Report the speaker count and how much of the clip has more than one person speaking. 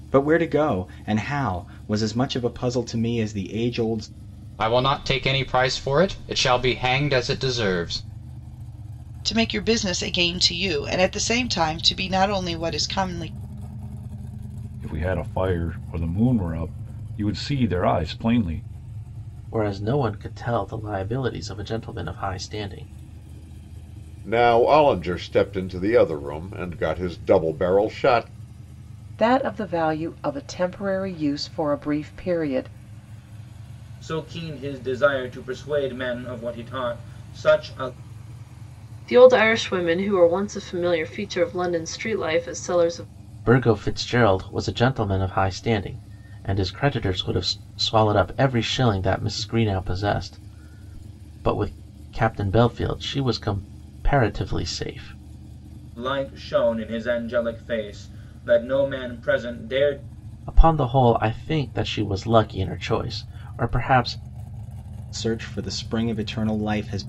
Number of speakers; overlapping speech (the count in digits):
9, no overlap